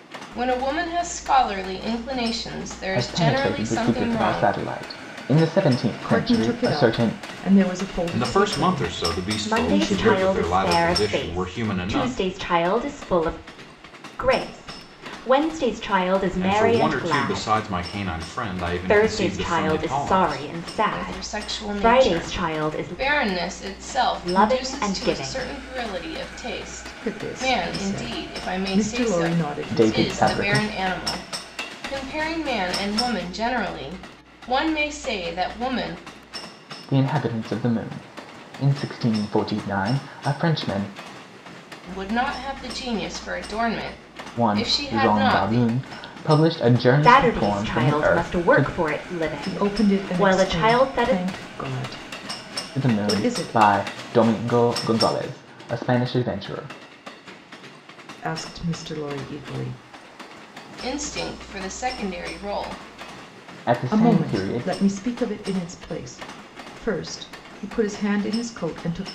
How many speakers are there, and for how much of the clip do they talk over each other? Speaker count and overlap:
5, about 33%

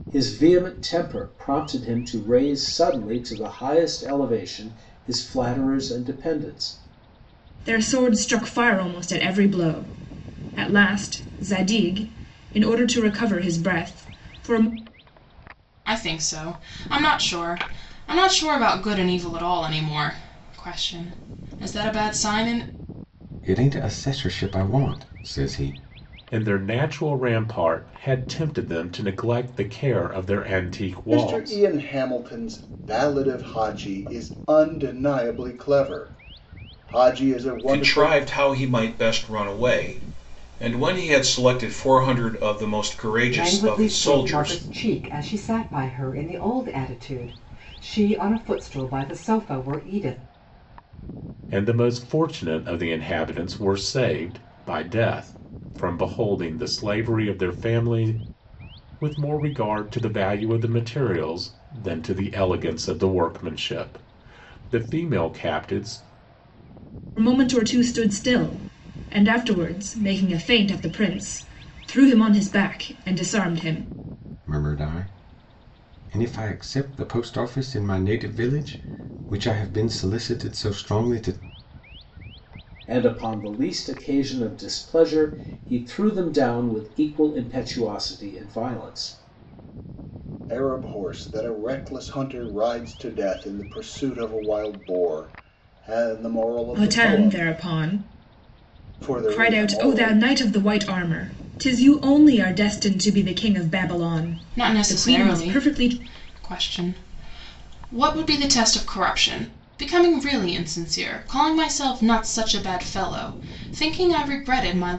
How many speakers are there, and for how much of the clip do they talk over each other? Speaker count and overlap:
8, about 5%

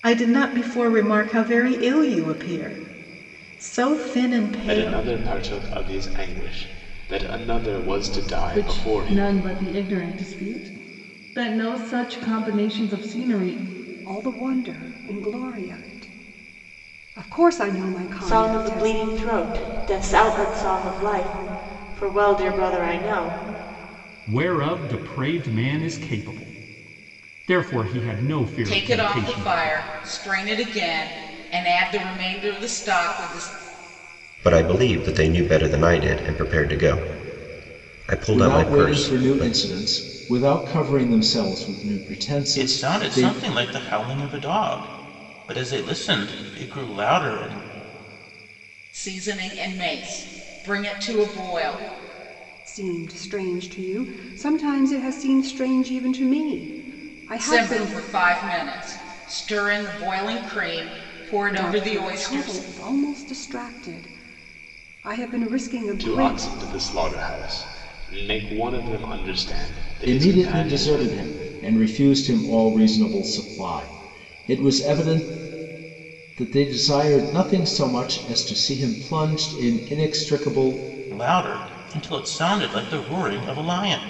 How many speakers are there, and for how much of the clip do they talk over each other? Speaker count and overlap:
10, about 10%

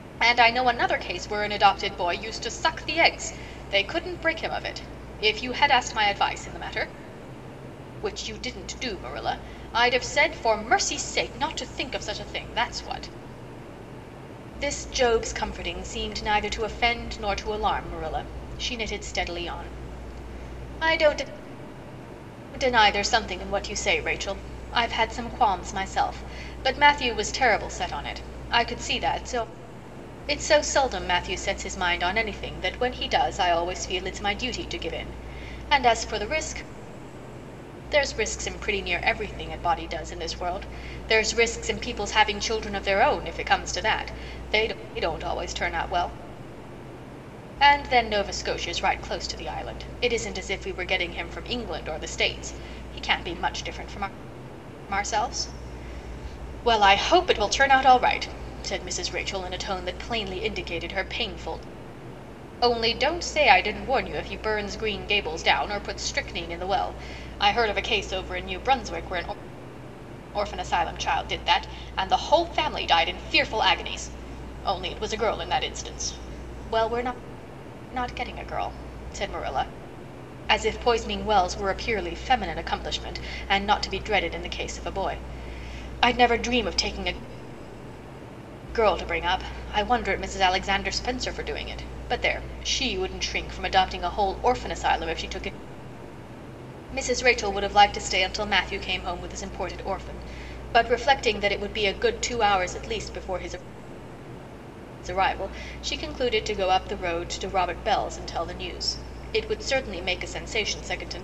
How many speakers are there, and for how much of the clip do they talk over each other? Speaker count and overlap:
1, no overlap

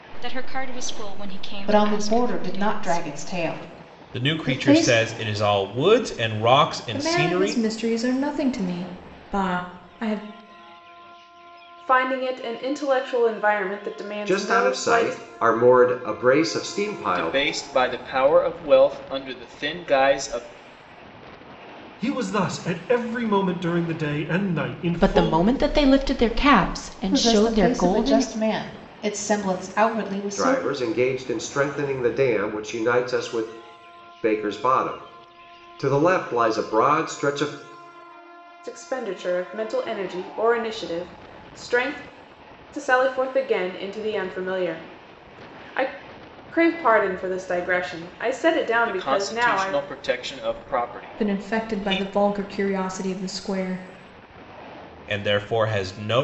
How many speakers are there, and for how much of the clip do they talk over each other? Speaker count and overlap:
9, about 15%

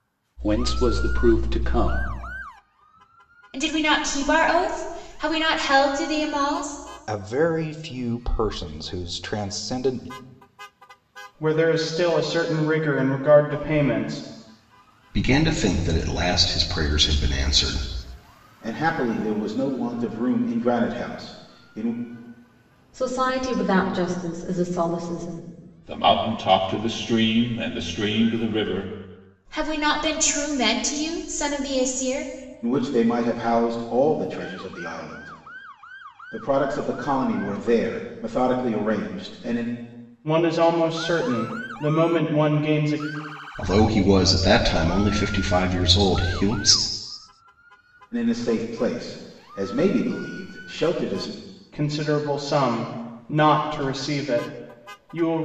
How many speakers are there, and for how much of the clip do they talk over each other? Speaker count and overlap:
8, no overlap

